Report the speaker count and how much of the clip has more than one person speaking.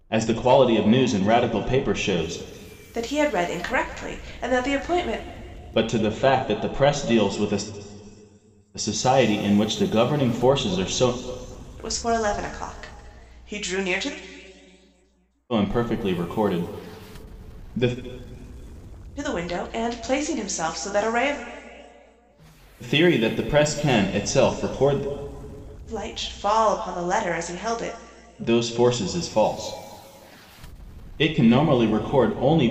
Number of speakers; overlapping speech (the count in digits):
2, no overlap